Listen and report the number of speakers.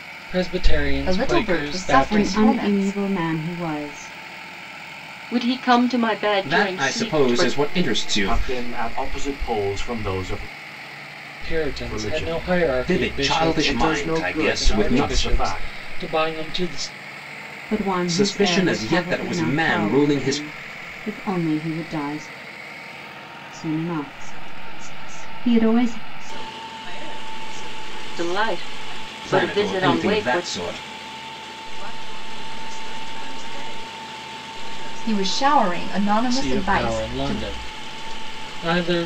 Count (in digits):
7